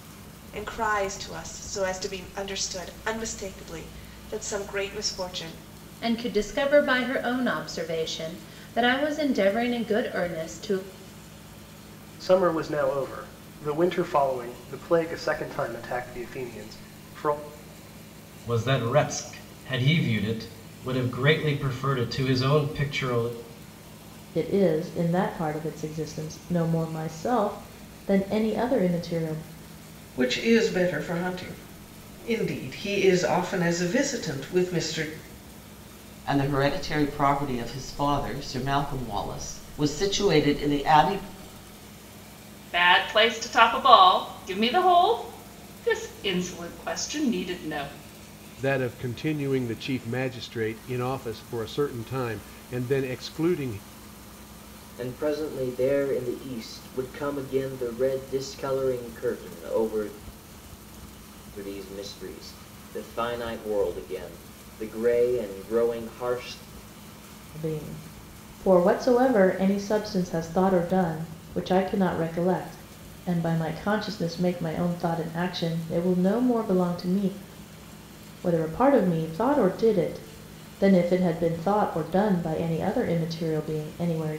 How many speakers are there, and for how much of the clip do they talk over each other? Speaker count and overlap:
10, no overlap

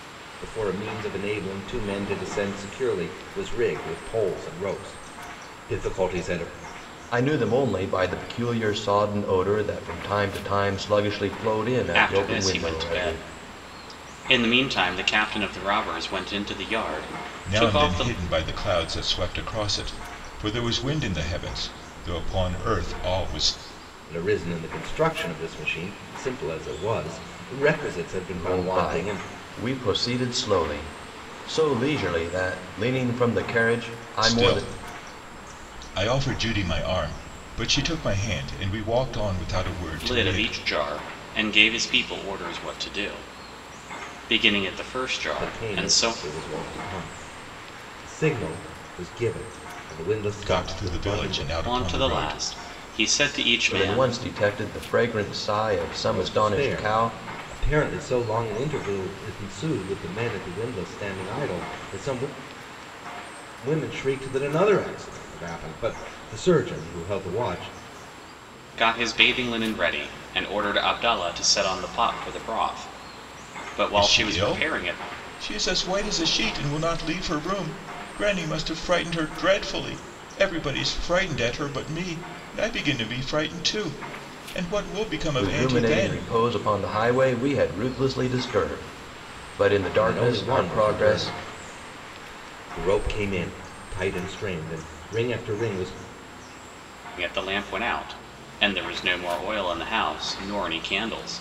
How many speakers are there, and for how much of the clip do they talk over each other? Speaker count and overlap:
4, about 11%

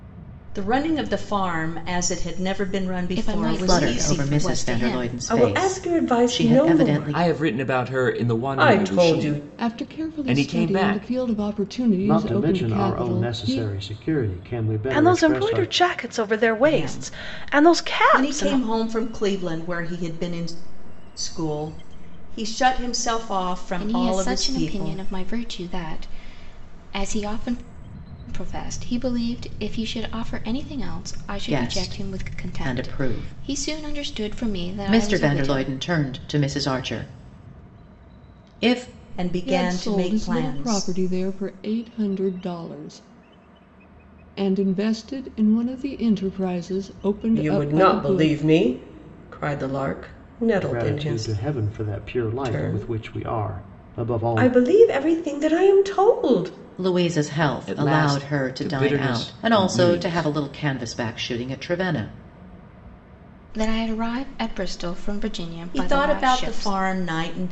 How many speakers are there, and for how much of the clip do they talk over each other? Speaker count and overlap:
8, about 38%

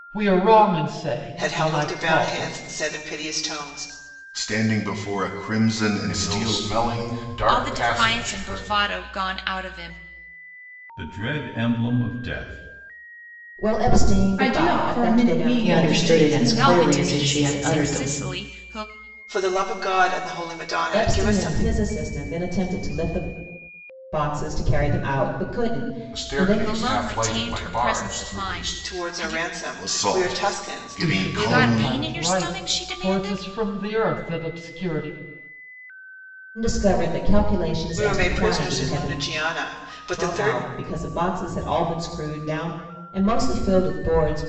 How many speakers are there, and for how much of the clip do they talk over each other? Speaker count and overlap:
9, about 37%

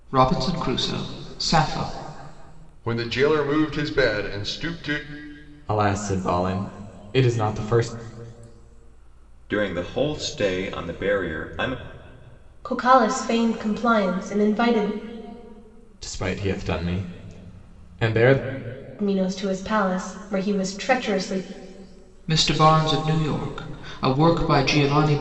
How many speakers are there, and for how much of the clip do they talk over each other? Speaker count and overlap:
5, no overlap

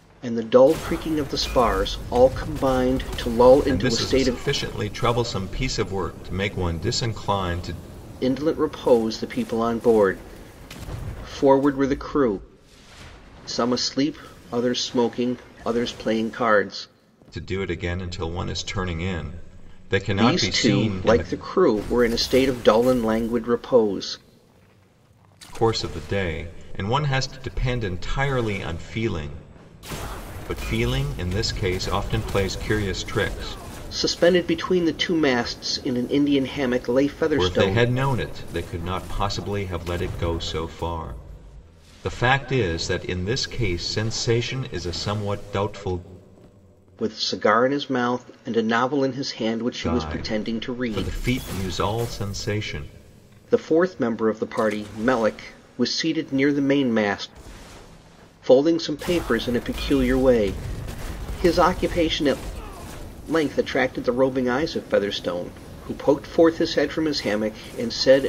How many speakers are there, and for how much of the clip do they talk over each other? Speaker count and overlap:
2, about 6%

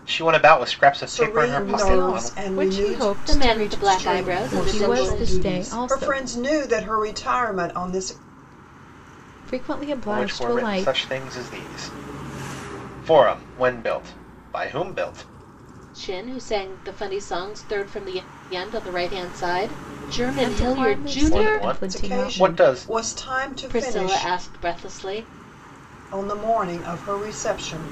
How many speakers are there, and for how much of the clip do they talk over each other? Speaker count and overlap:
4, about 33%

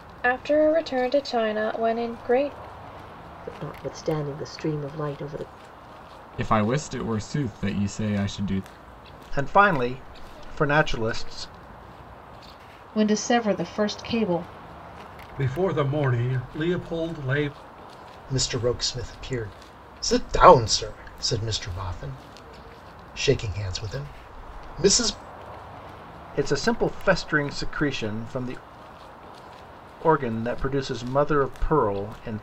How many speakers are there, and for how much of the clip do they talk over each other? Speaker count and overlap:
7, no overlap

